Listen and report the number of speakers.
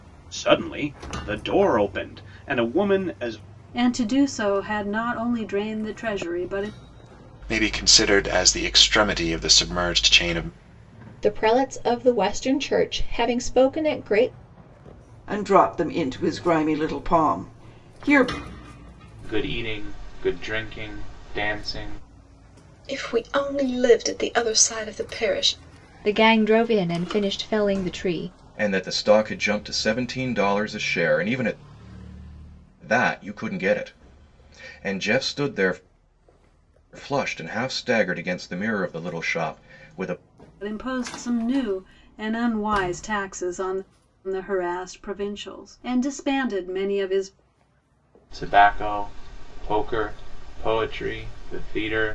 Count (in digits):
9